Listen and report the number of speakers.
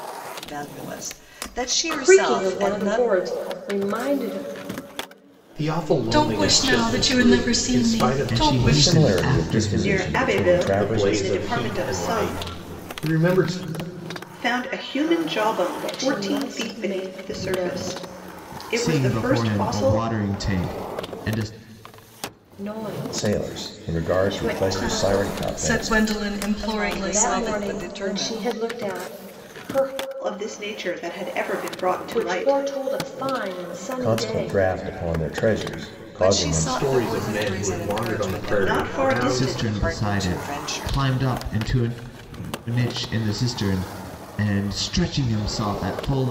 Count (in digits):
7